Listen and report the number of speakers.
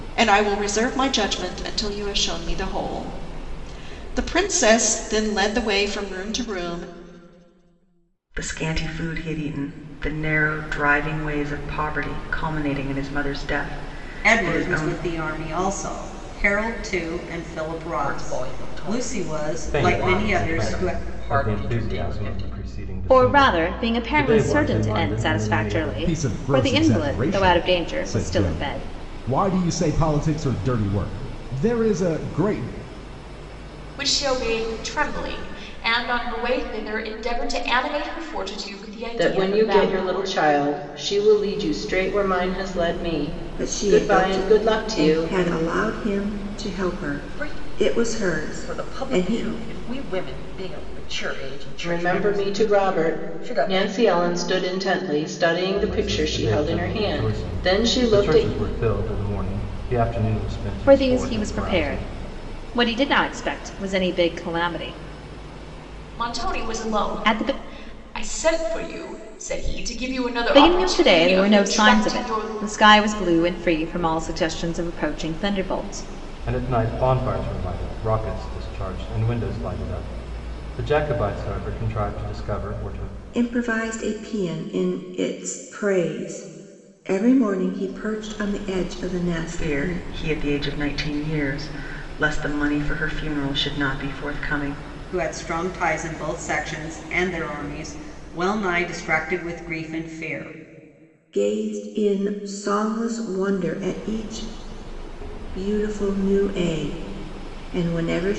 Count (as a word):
ten